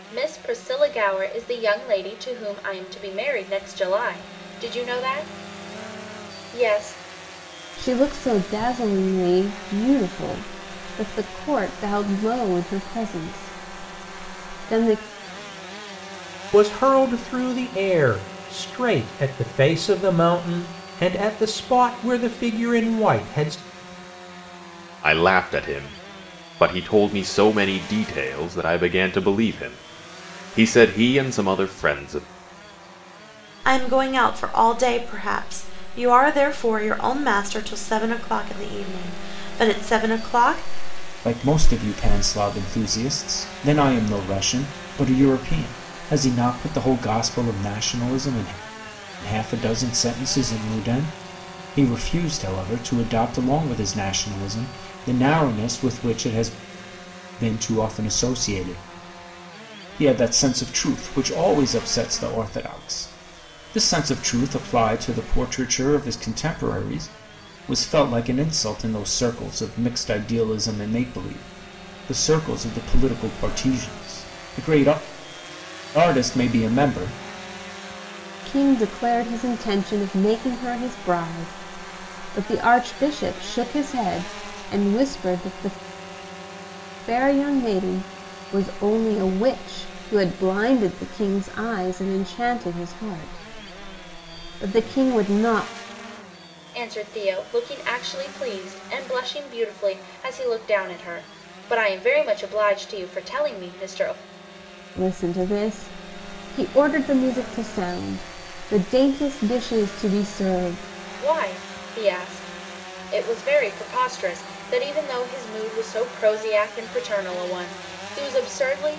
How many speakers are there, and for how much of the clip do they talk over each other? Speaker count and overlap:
6, no overlap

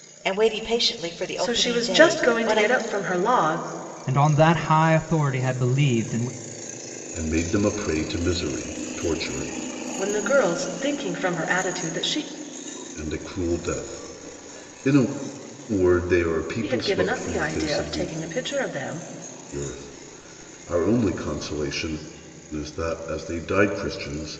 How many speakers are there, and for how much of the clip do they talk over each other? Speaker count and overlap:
4, about 11%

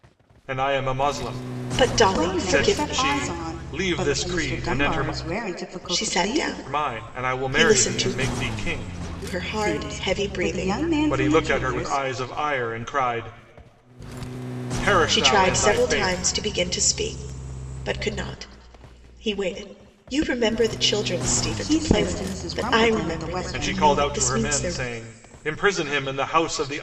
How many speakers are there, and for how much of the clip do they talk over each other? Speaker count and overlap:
3, about 46%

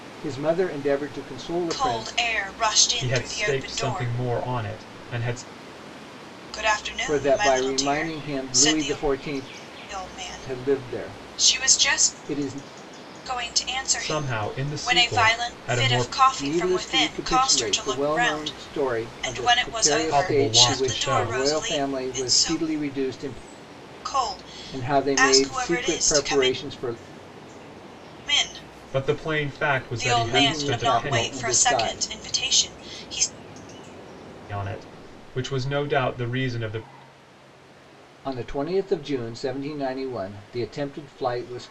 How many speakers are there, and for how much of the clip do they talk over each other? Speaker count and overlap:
3, about 46%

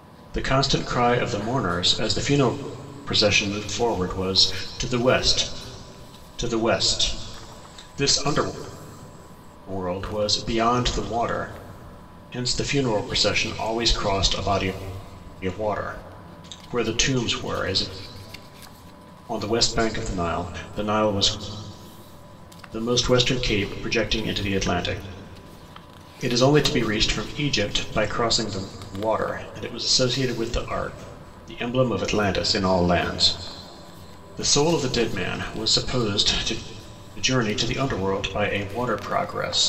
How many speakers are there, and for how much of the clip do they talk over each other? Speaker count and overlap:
1, no overlap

